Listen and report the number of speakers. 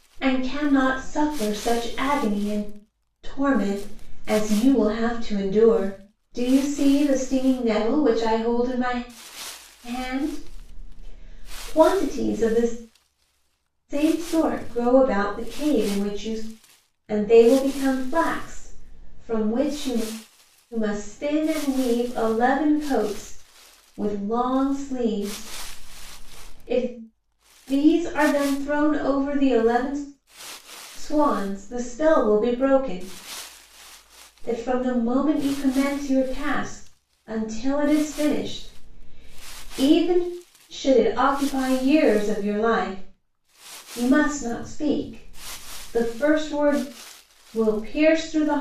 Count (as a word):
one